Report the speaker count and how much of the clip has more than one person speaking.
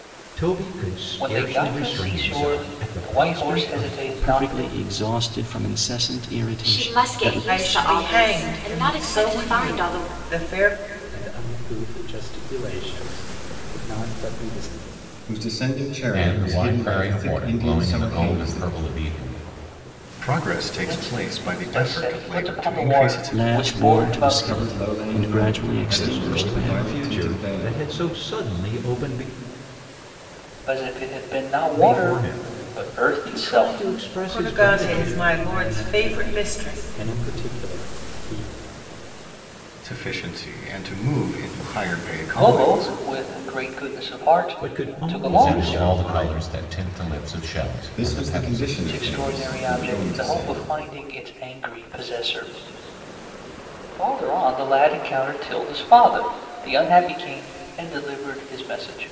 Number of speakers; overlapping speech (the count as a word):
nine, about 45%